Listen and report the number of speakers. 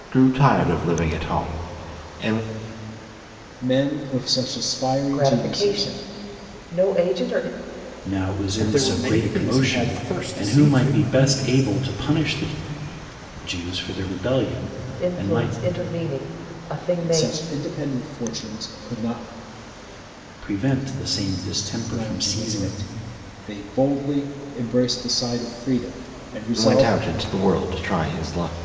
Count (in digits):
5